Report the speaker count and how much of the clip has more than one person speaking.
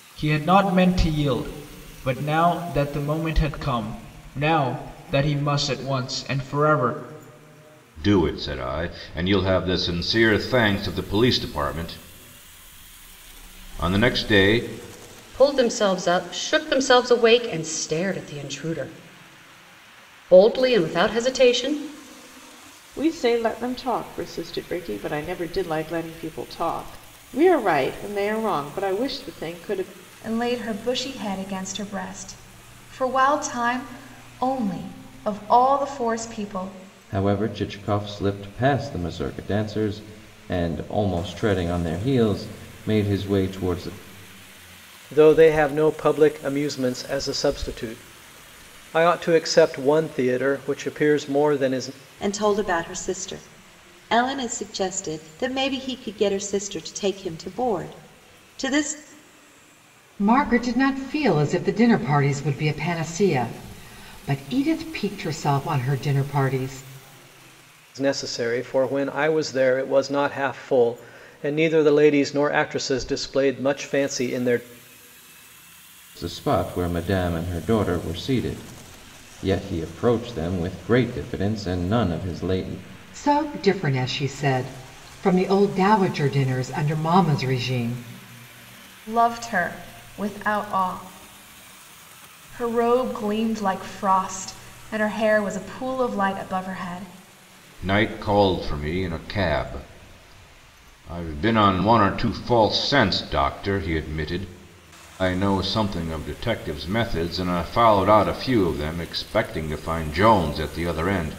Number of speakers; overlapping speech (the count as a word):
nine, no overlap